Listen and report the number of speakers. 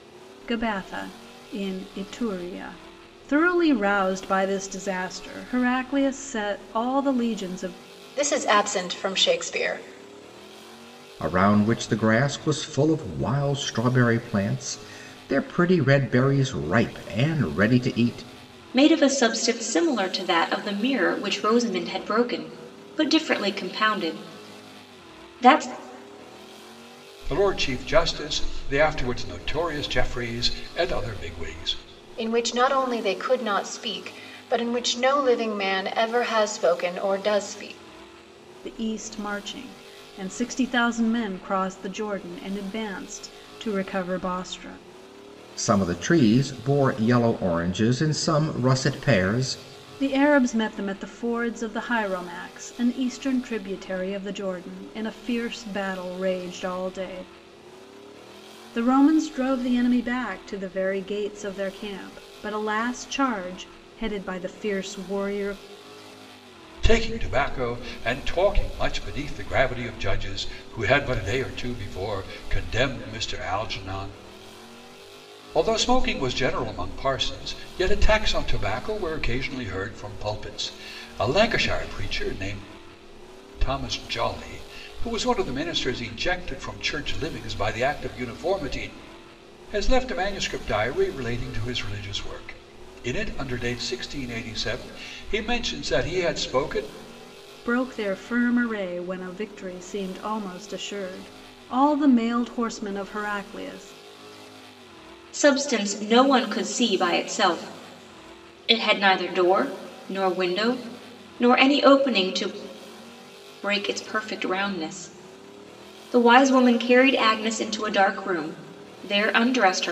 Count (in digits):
5